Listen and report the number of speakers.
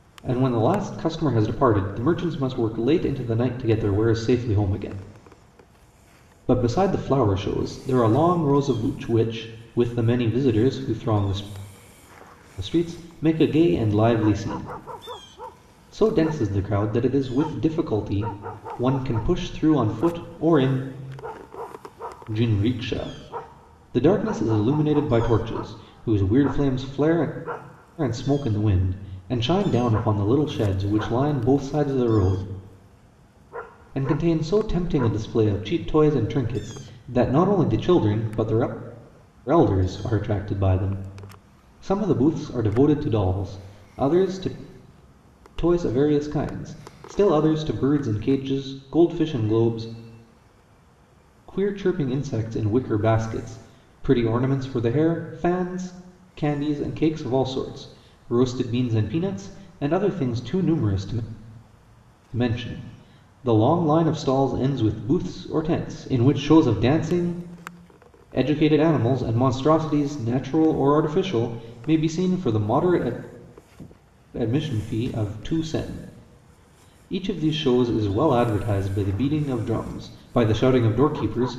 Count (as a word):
one